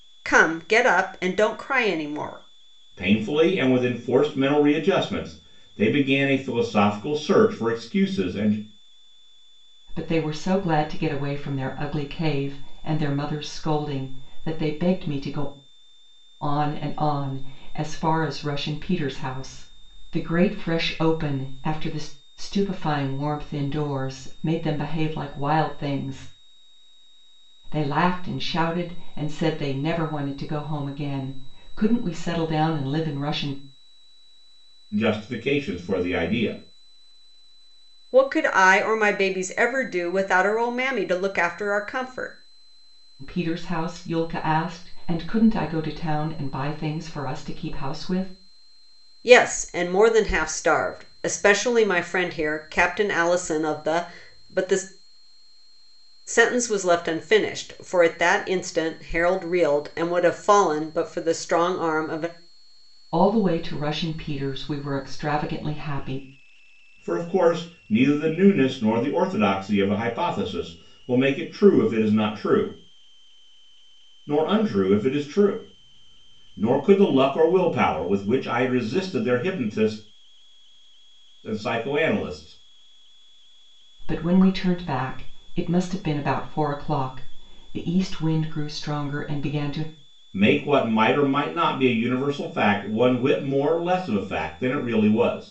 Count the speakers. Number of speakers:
three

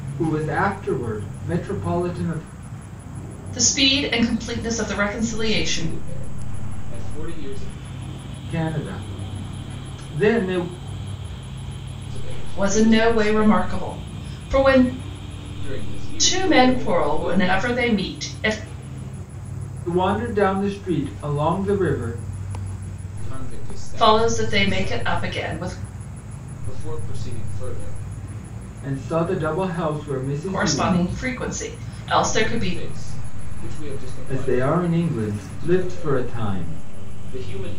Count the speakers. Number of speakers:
three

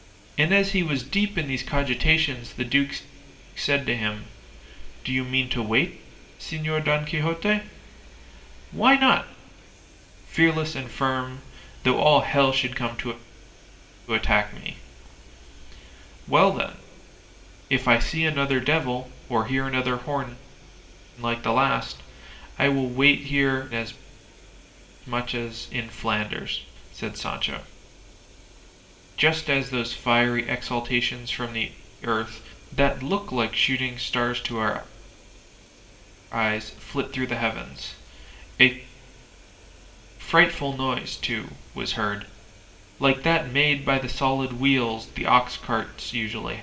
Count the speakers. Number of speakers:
one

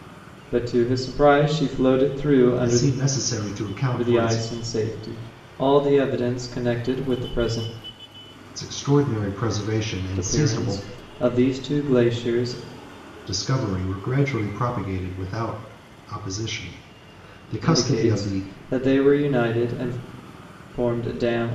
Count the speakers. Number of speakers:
two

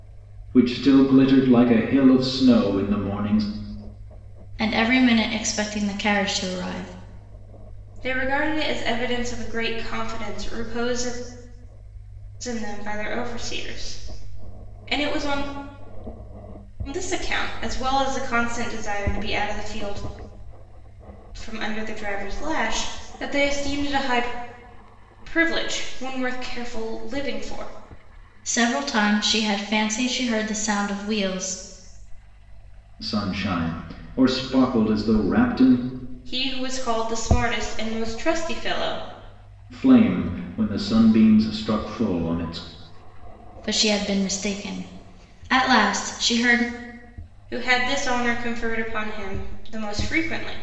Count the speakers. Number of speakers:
three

